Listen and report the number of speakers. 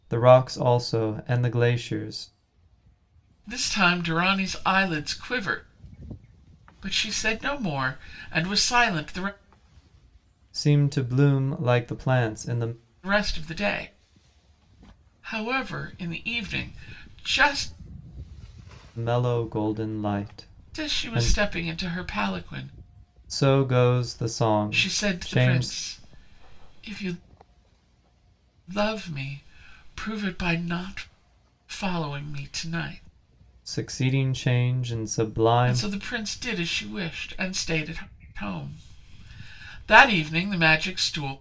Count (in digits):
2